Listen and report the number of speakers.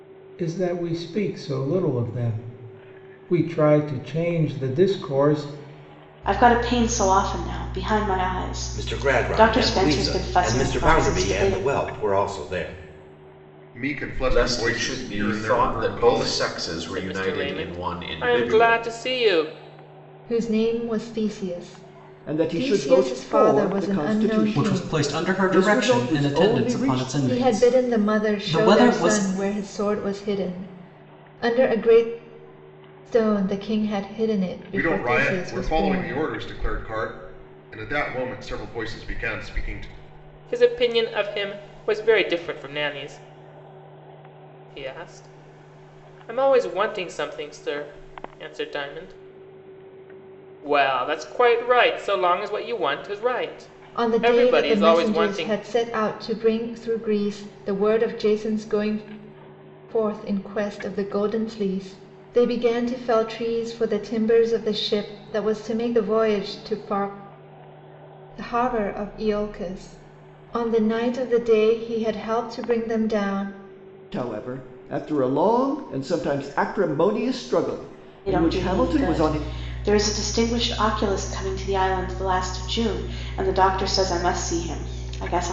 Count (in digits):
9